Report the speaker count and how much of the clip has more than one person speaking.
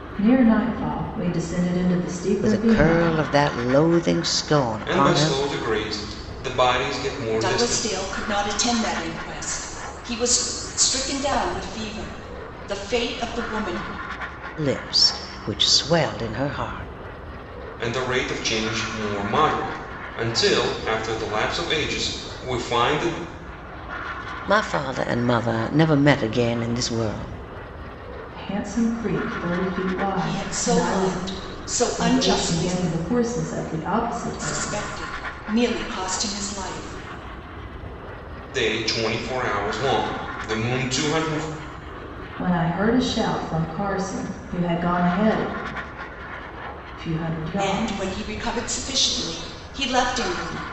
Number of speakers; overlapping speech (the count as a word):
four, about 9%